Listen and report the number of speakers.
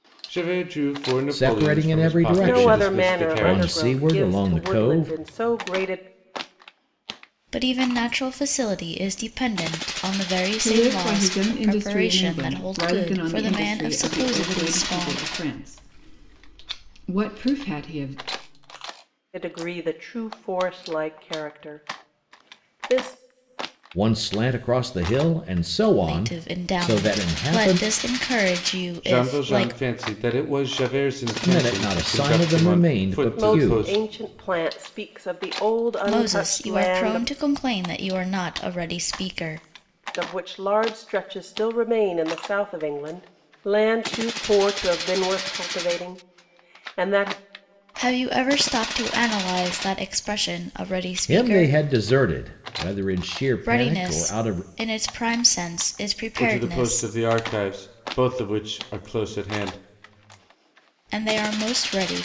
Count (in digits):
5